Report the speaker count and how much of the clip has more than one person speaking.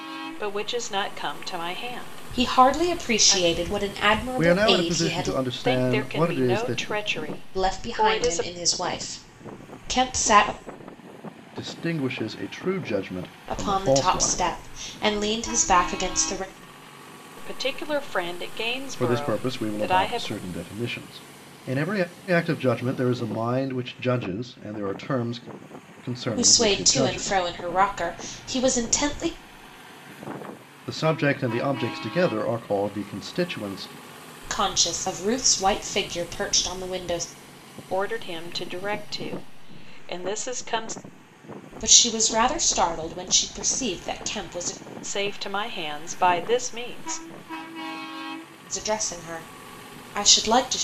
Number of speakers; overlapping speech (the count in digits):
3, about 16%